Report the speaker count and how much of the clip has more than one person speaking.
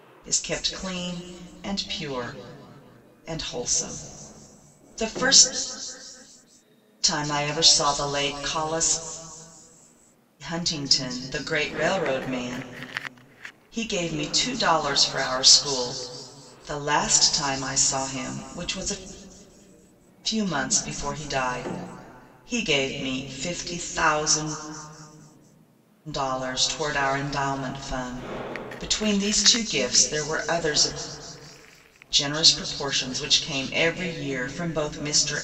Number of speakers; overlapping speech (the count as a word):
one, no overlap